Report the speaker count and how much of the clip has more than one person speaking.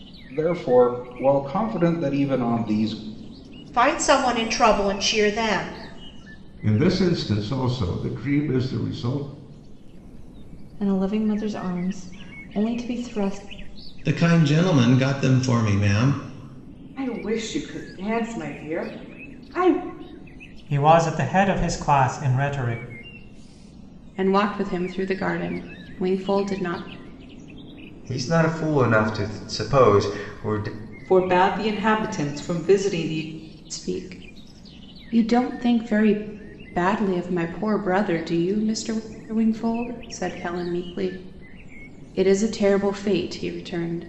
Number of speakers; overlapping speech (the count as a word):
ten, no overlap